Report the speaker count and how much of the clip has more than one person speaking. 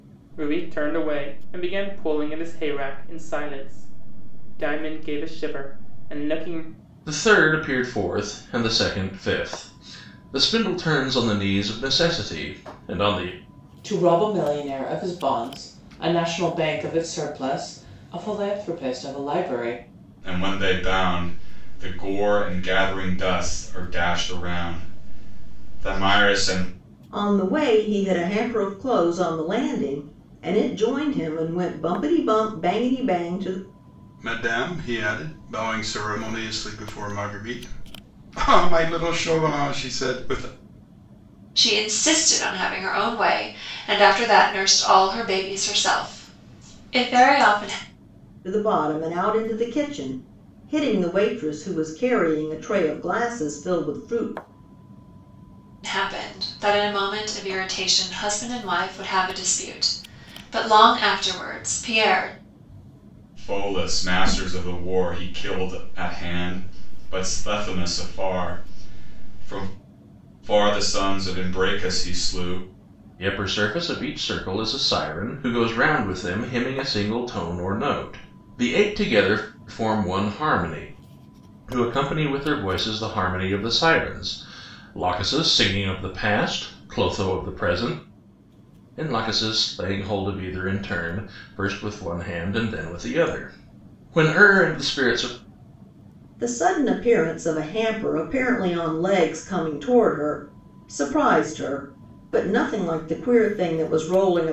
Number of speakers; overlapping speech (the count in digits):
7, no overlap